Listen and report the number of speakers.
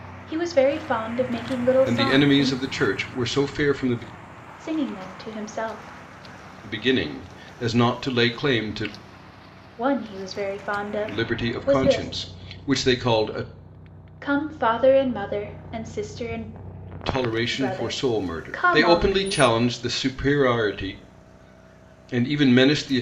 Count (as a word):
two